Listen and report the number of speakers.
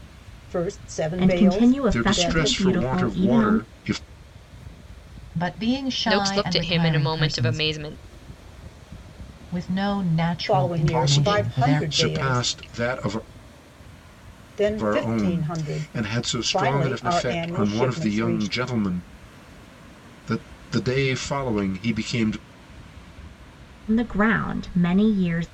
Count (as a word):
five